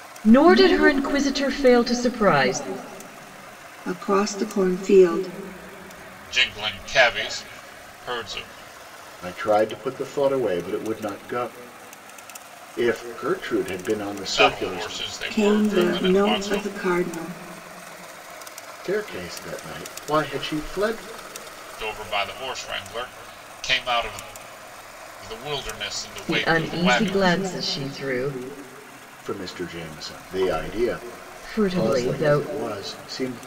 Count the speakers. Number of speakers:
four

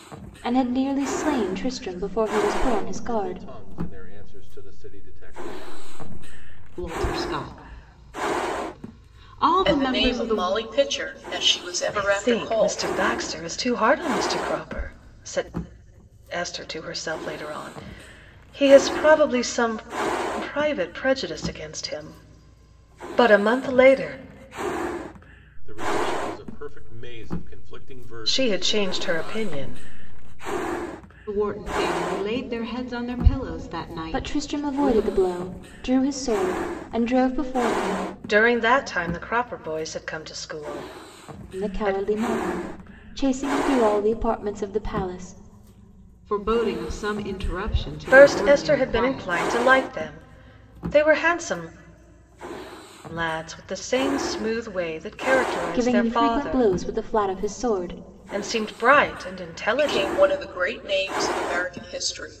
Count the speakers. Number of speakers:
five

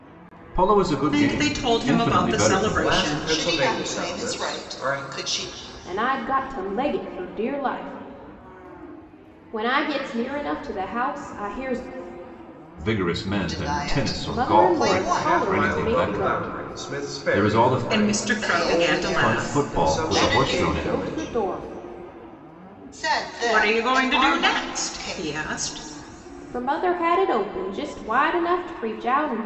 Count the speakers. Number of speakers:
five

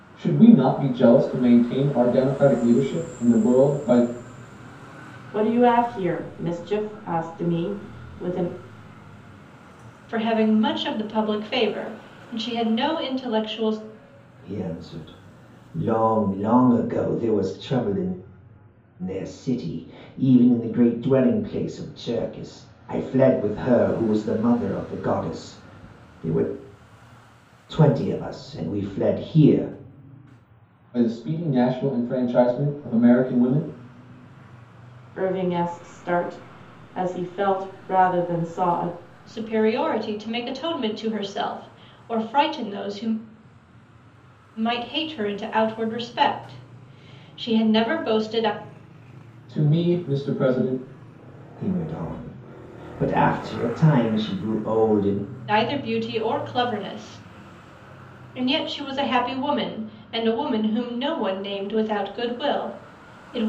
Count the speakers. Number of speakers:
four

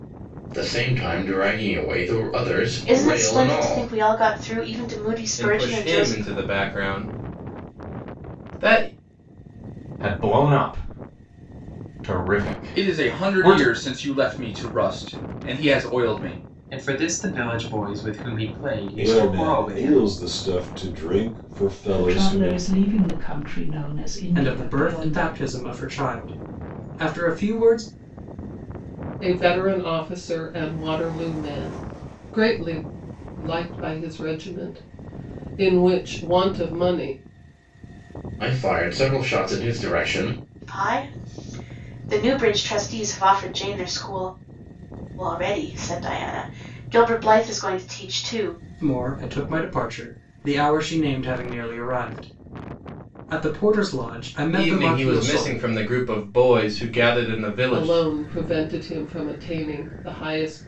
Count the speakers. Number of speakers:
ten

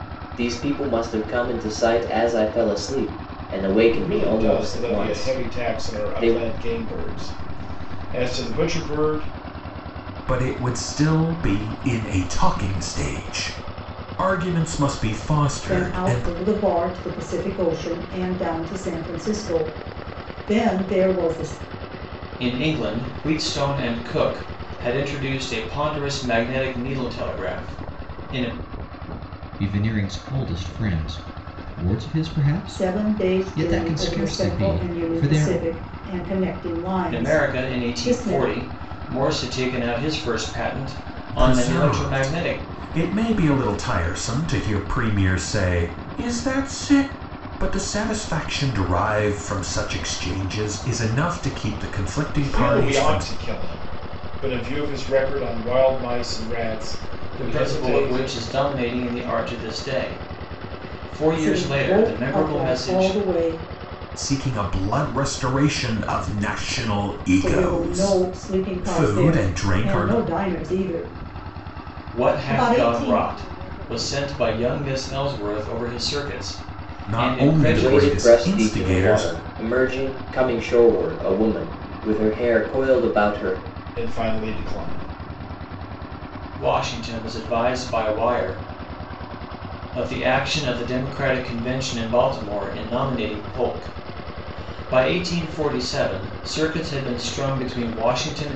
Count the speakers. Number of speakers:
six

